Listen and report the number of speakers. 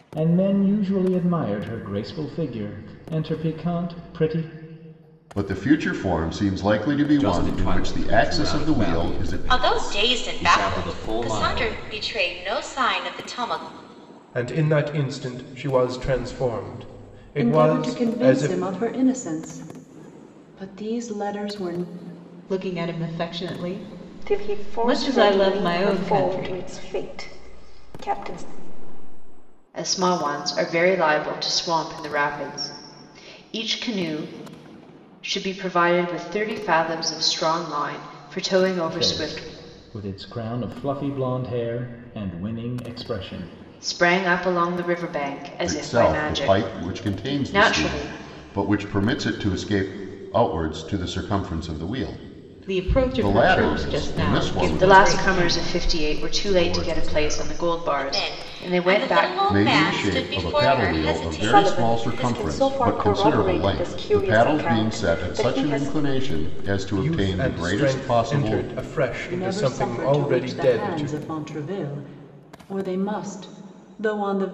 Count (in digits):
9